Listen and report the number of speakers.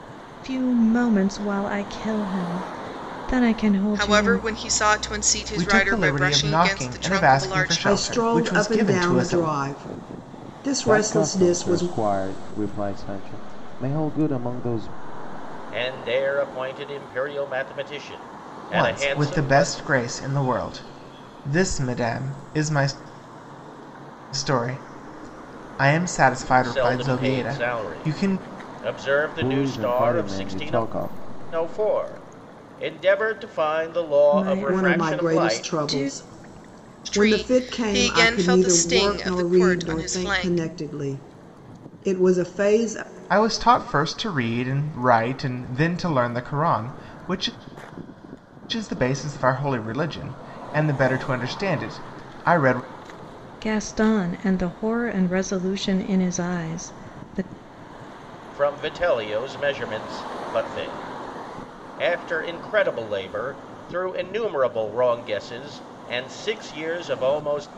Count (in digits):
6